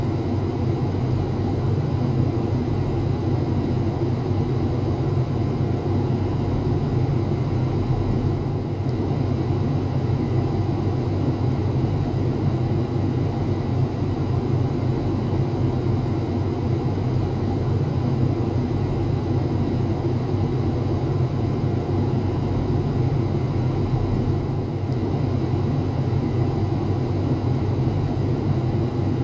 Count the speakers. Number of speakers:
zero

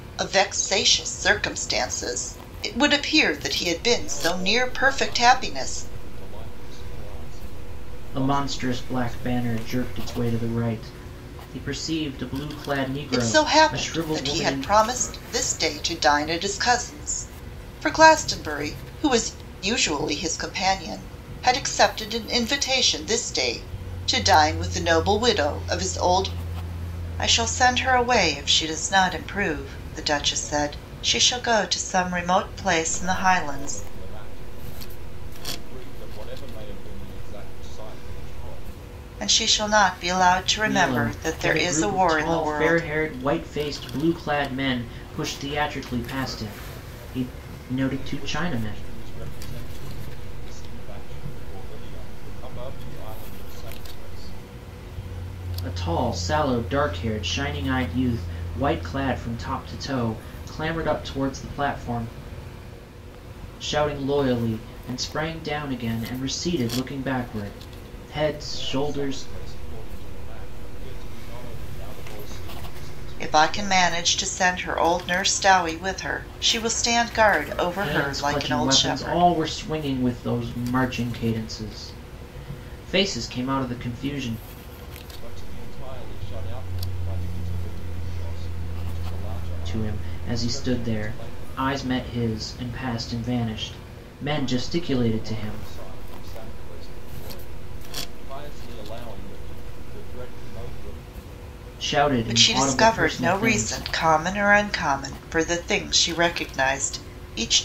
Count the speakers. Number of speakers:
three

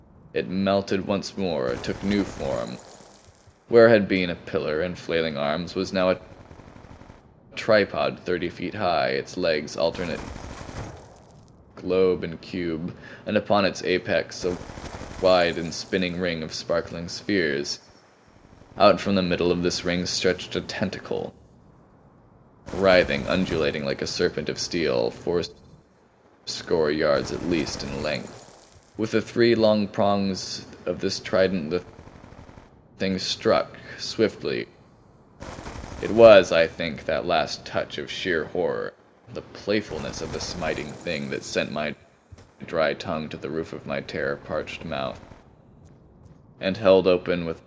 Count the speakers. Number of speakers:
one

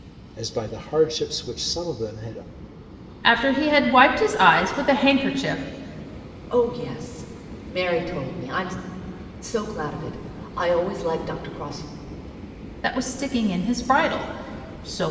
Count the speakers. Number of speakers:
three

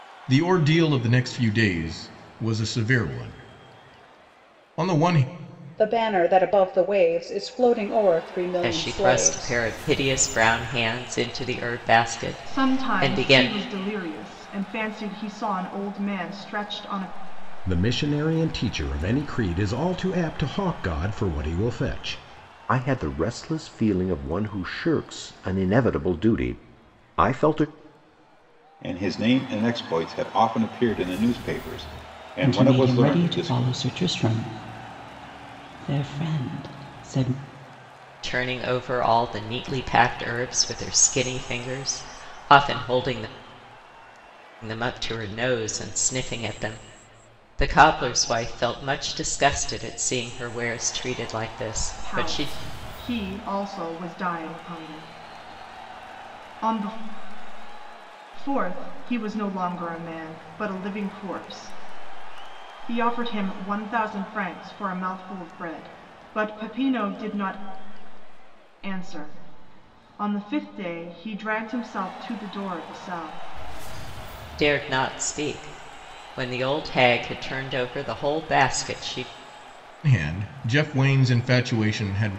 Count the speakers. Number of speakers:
eight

